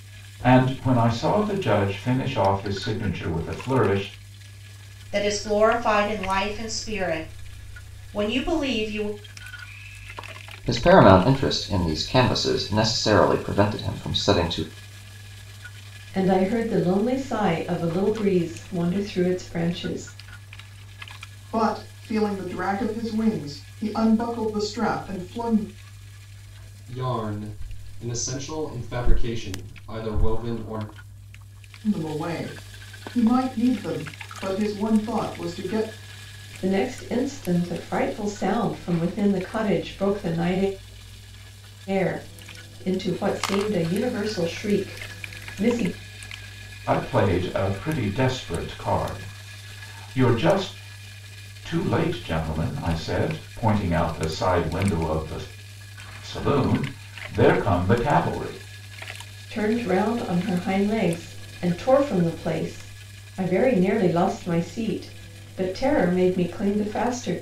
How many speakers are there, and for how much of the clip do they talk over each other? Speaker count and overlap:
6, no overlap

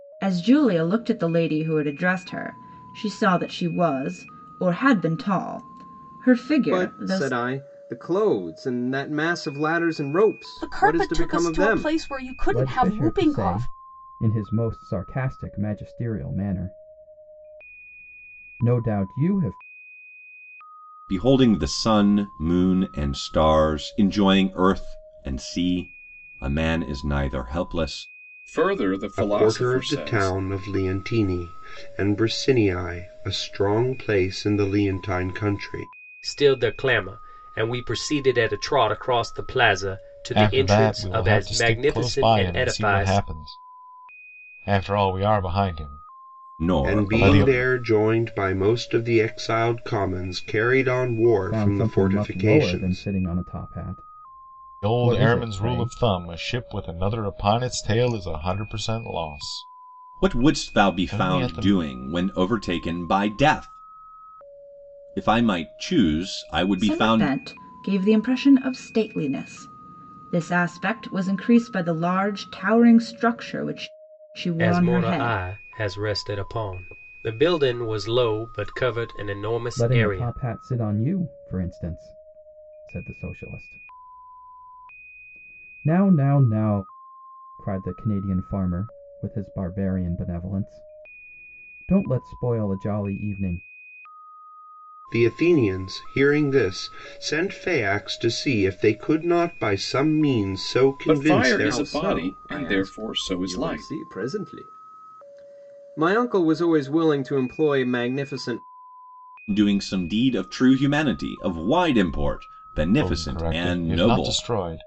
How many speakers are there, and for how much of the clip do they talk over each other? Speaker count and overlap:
9, about 17%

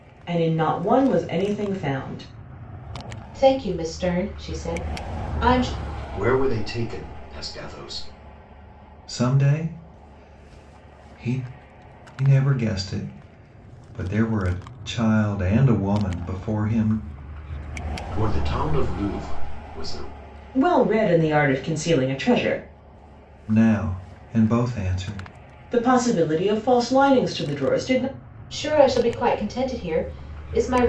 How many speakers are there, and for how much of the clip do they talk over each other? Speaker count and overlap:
4, no overlap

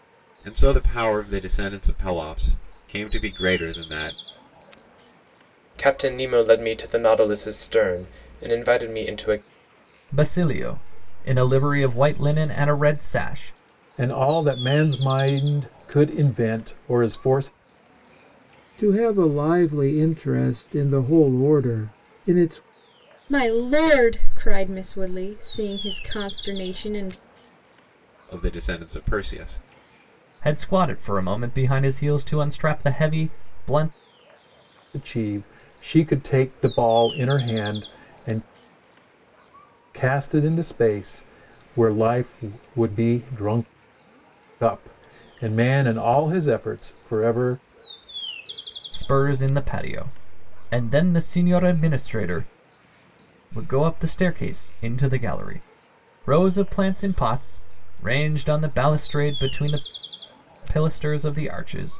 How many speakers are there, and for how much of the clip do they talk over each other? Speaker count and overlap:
6, no overlap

